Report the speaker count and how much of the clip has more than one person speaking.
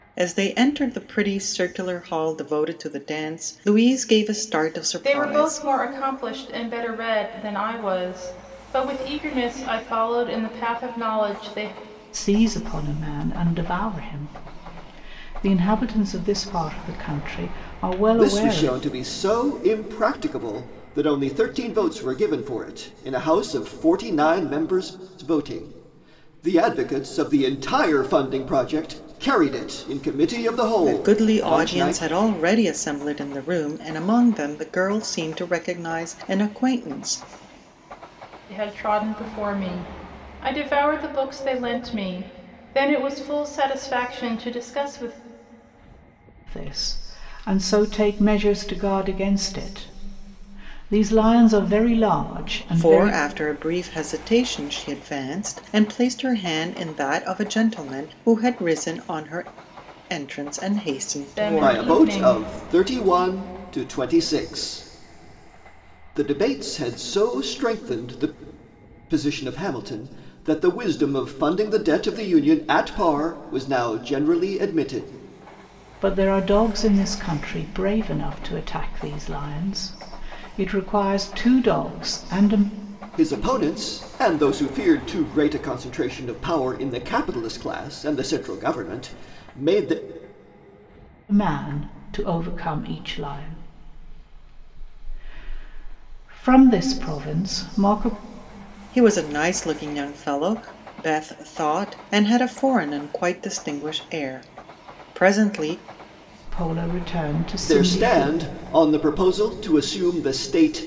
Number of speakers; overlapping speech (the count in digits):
4, about 4%